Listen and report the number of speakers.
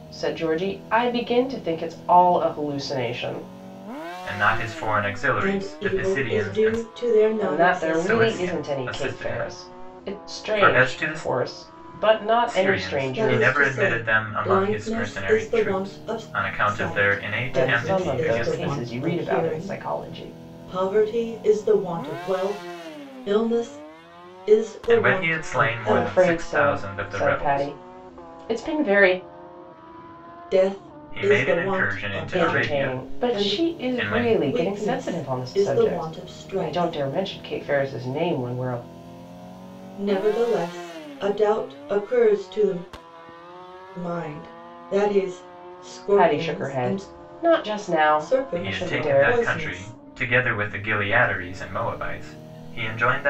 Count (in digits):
3